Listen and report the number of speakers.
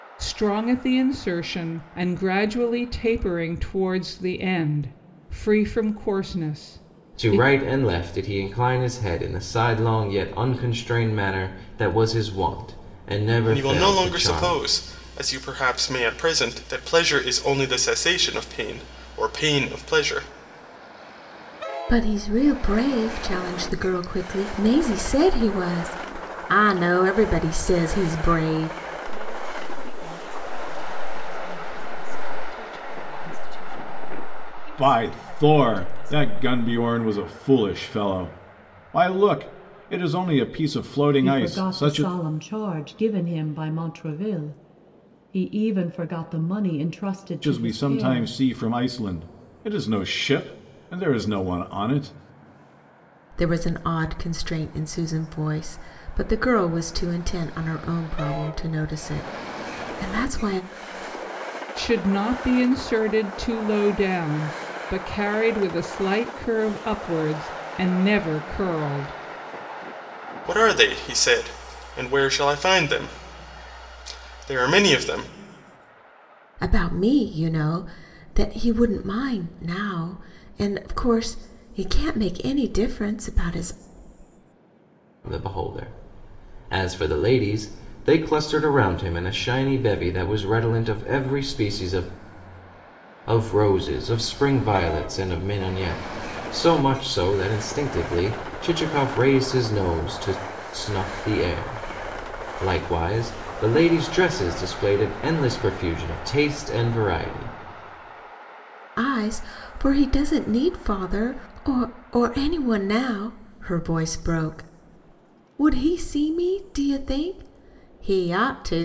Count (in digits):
7